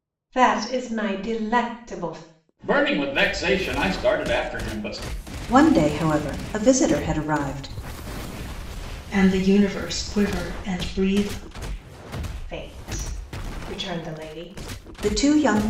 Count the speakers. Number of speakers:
four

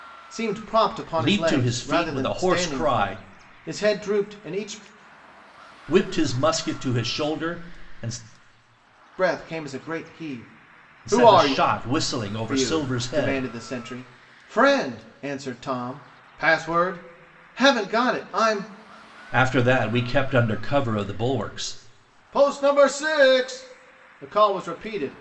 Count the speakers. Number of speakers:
two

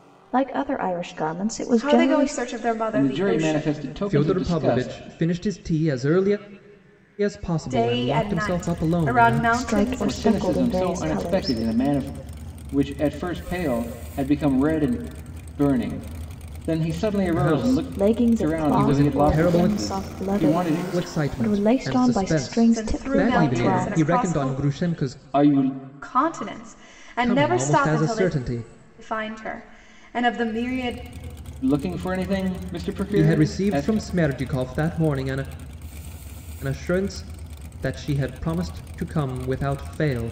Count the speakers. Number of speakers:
four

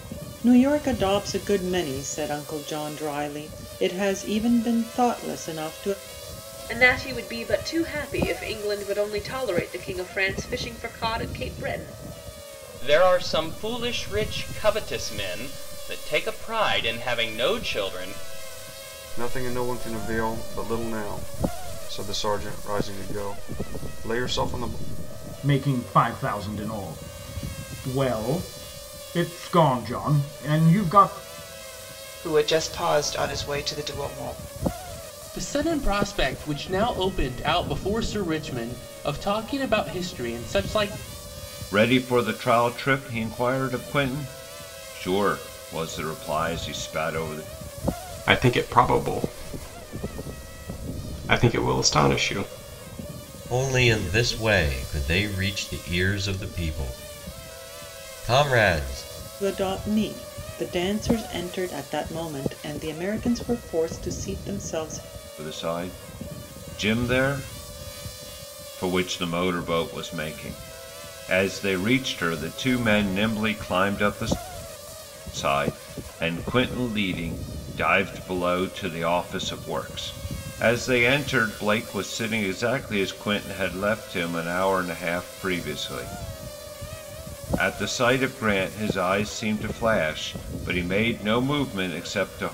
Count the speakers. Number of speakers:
ten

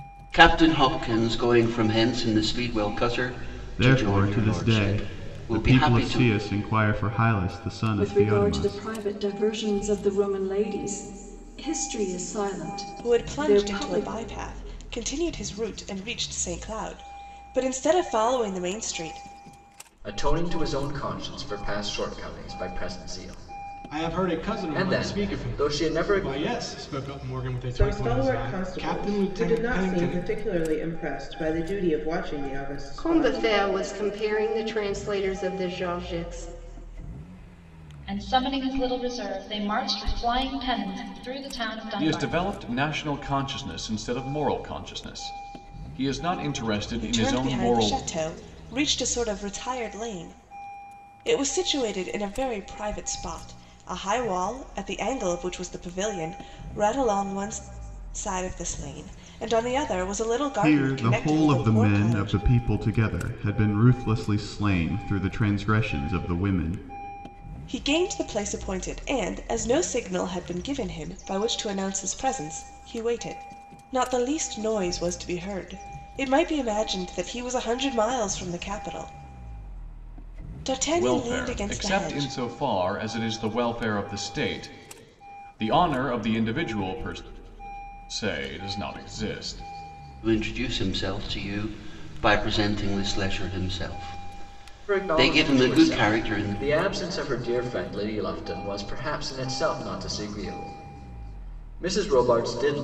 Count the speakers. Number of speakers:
ten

